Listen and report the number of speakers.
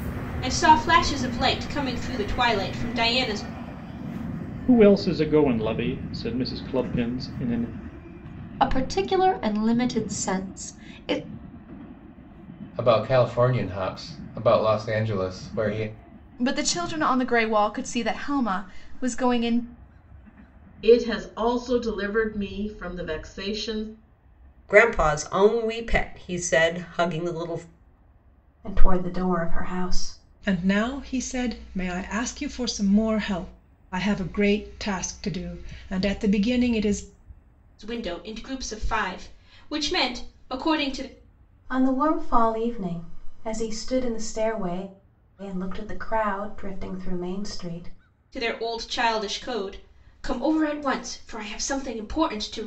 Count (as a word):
nine